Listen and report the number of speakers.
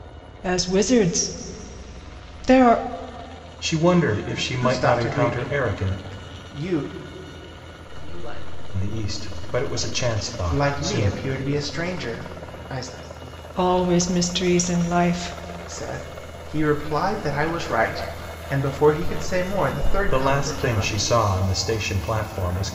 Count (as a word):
four